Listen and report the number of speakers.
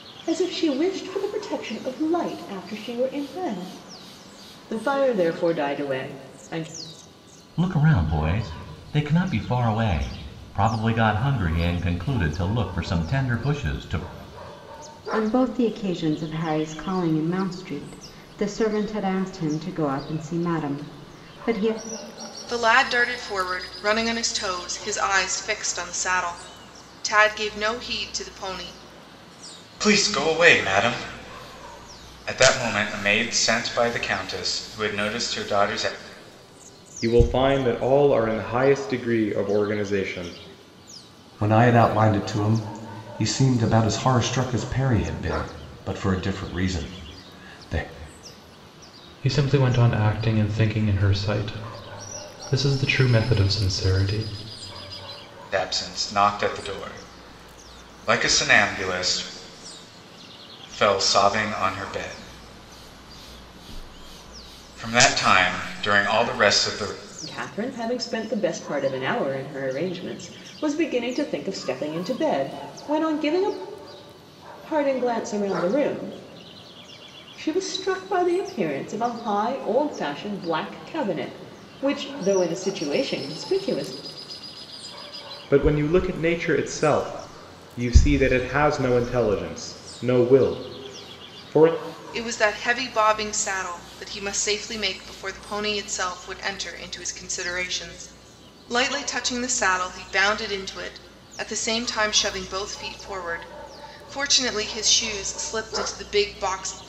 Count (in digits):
8